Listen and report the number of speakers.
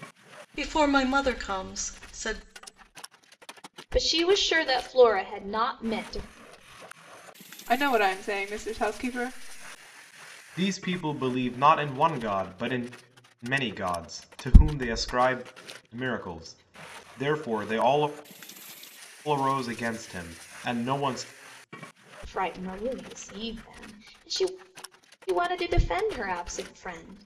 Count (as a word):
four